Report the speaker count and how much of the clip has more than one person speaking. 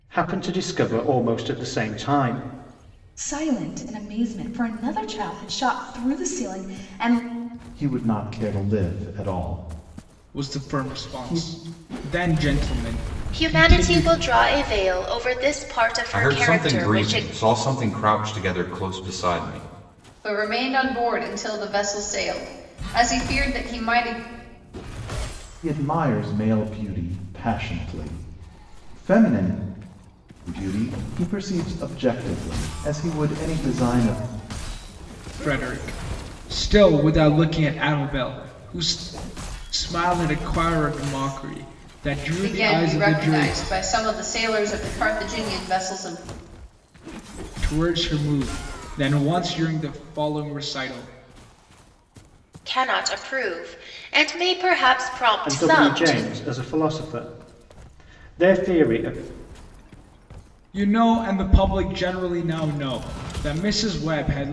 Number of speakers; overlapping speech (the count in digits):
7, about 8%